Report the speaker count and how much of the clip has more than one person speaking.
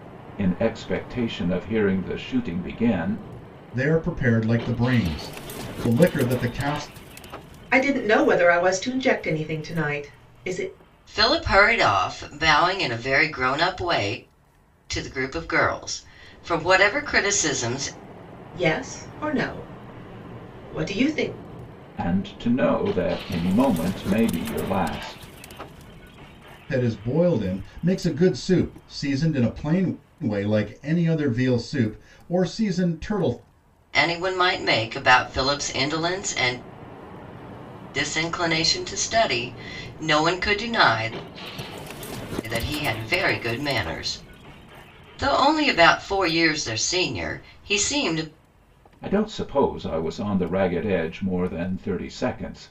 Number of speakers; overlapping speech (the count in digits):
4, no overlap